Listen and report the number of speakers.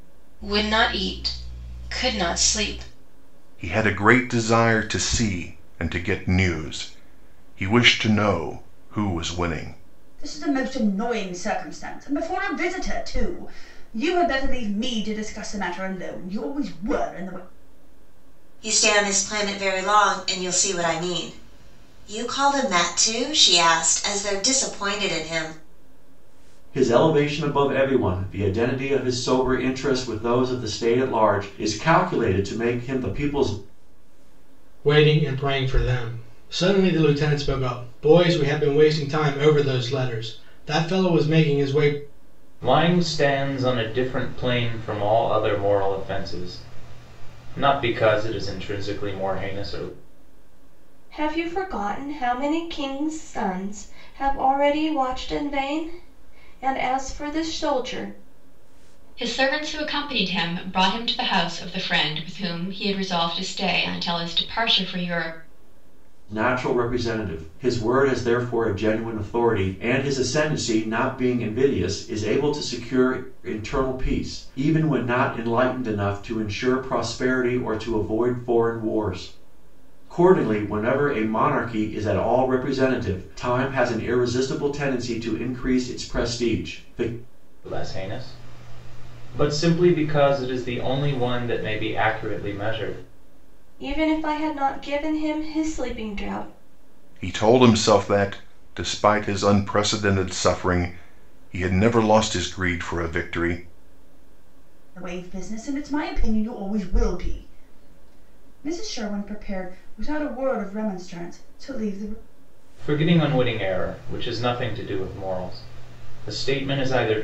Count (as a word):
nine